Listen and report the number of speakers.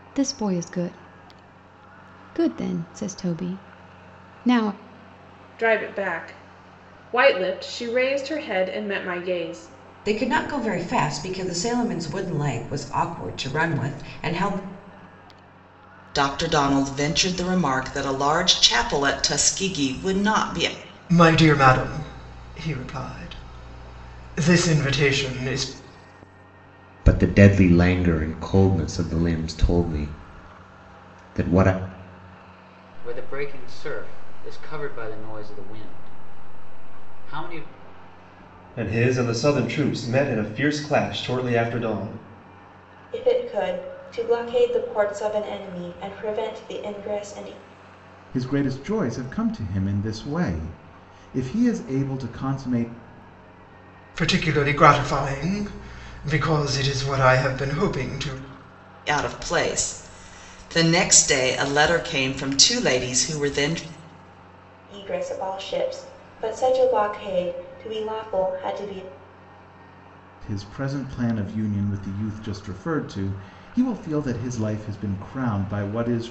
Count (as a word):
ten